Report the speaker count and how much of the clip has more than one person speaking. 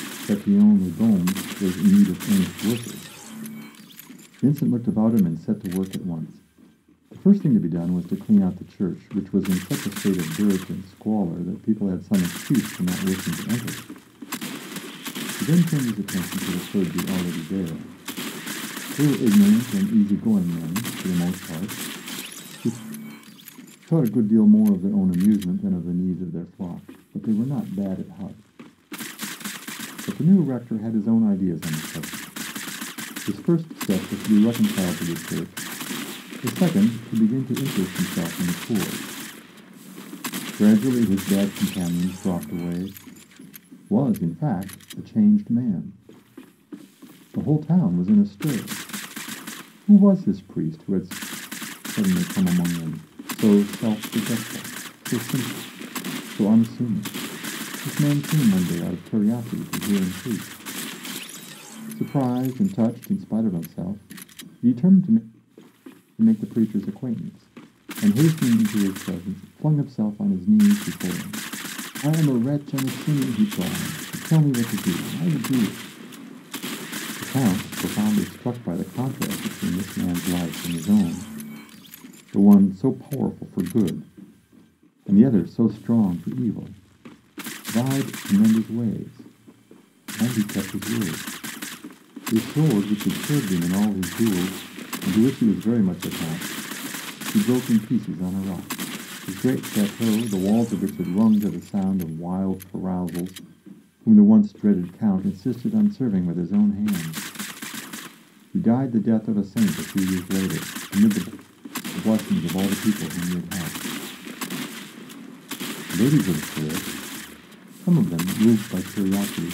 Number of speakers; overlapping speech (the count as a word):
one, no overlap